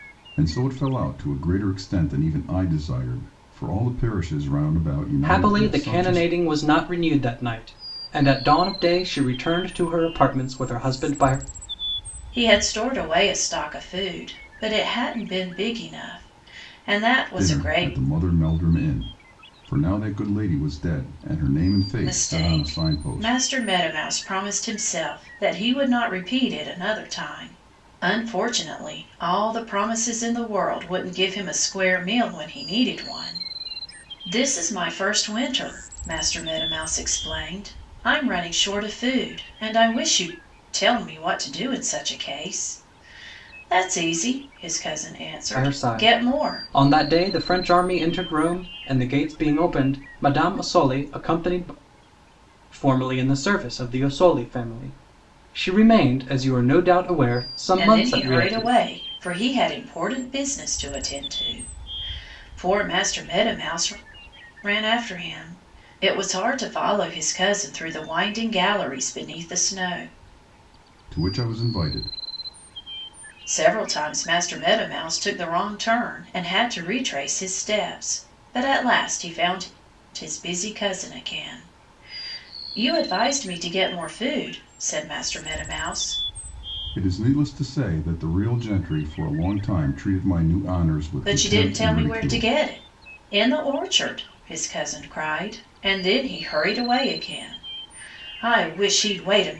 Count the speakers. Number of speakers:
3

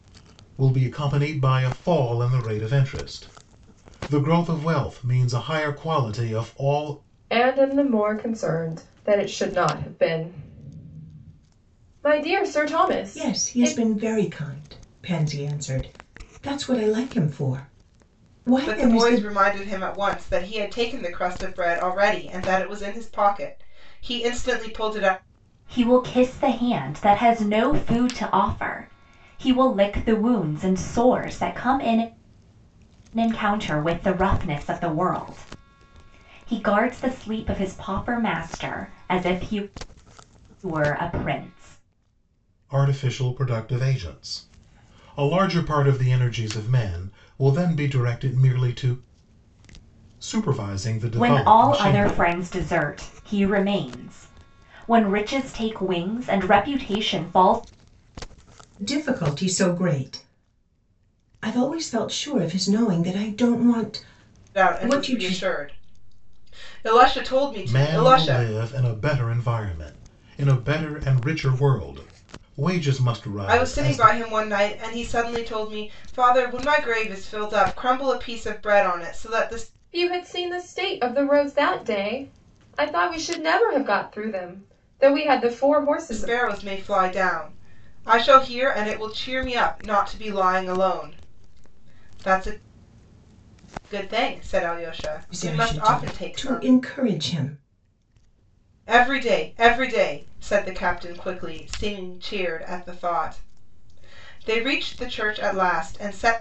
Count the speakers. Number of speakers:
5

